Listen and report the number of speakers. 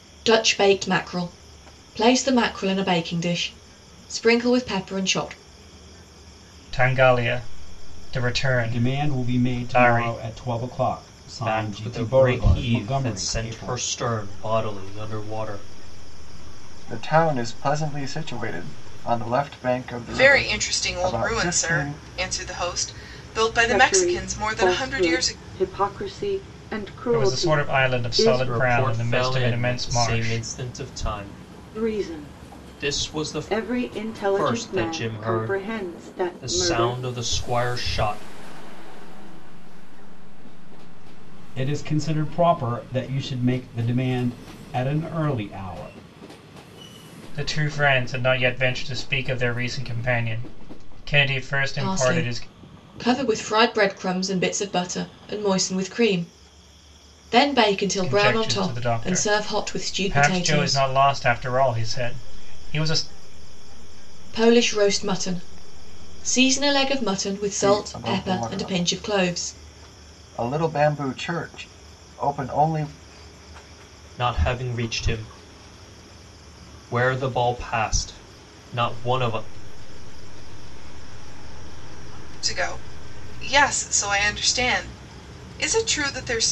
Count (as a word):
eight